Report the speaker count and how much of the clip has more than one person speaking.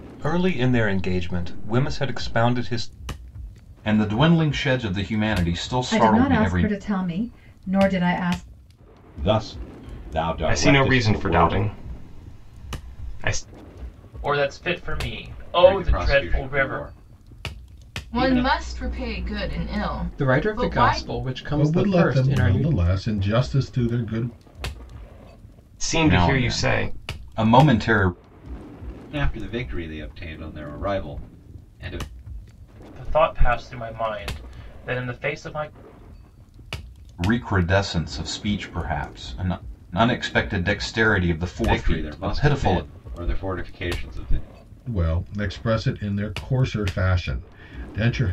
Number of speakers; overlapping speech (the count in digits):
10, about 16%